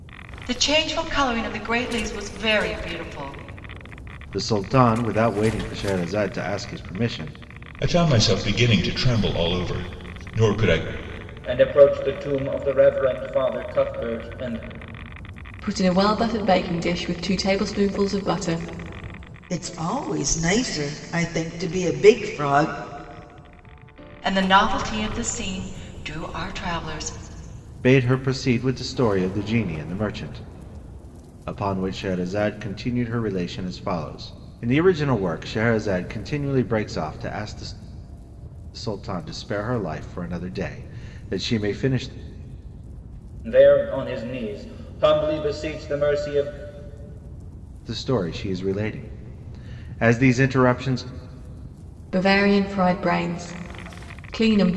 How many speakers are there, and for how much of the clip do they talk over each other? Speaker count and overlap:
six, no overlap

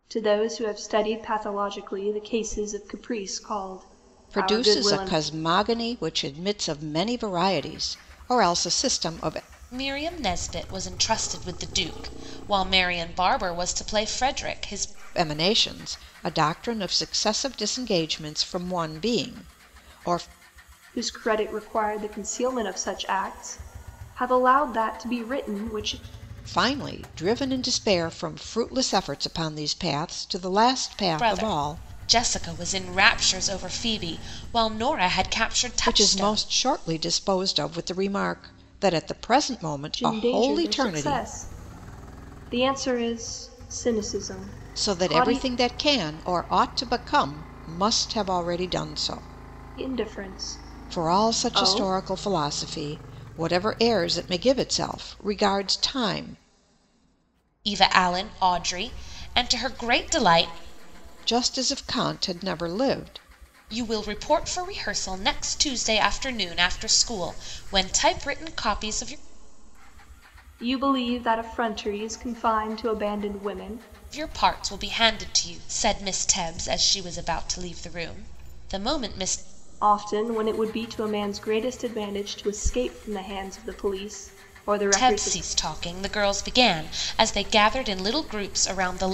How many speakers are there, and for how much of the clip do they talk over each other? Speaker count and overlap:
three, about 7%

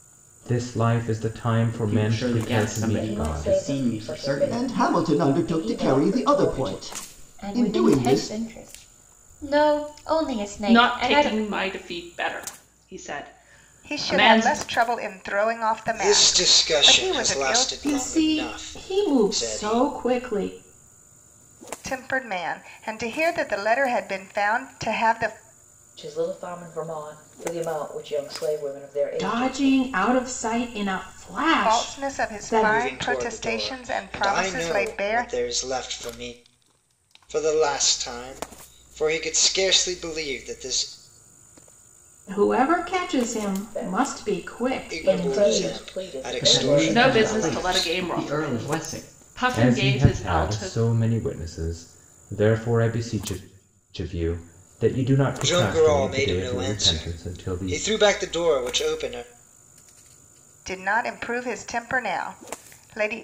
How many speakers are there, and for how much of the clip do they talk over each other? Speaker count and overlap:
nine, about 39%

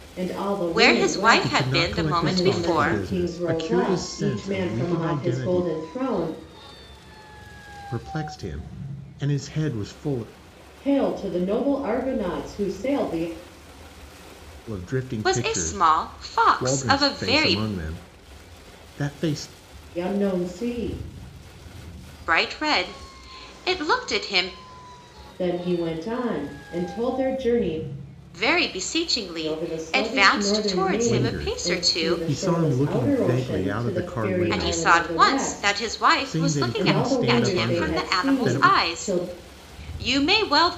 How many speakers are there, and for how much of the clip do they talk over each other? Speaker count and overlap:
three, about 41%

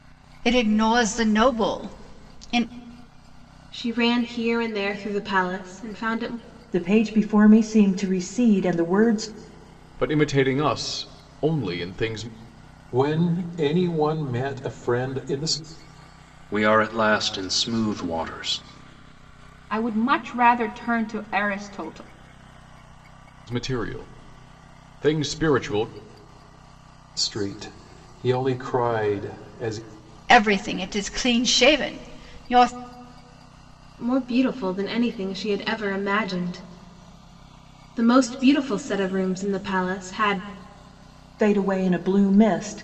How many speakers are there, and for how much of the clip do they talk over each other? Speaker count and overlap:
seven, no overlap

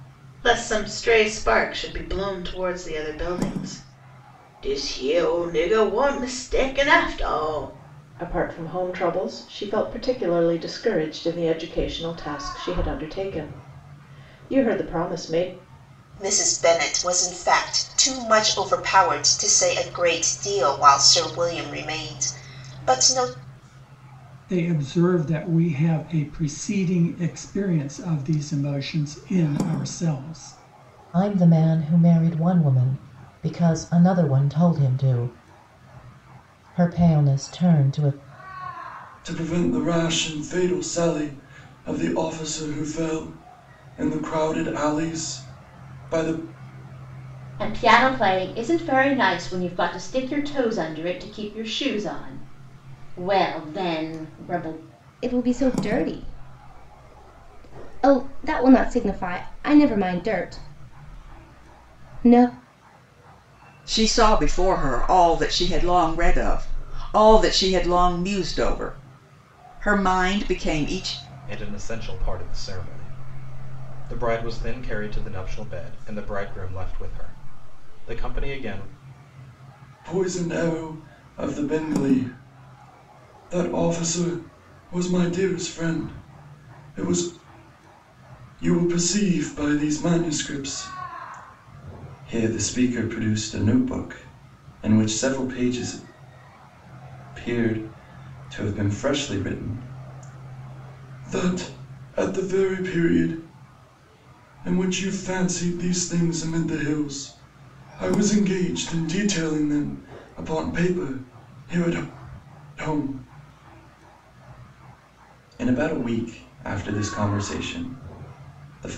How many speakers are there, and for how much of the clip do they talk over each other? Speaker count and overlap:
ten, no overlap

